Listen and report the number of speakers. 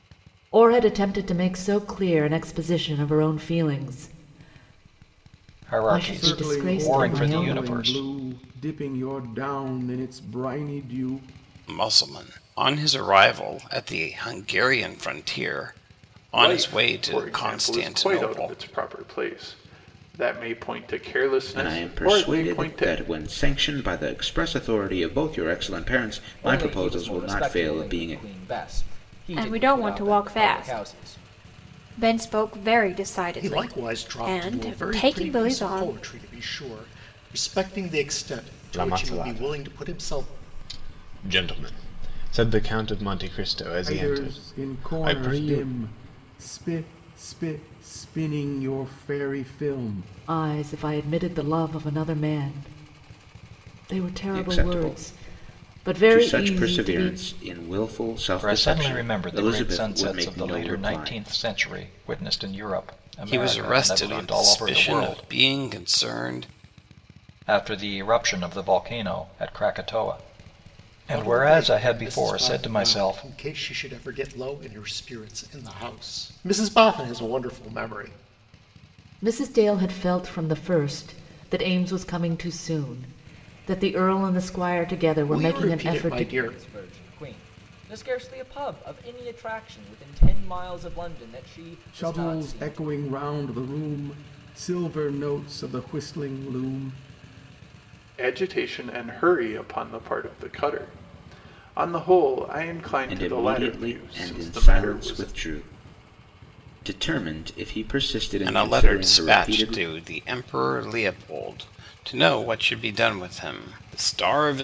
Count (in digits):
10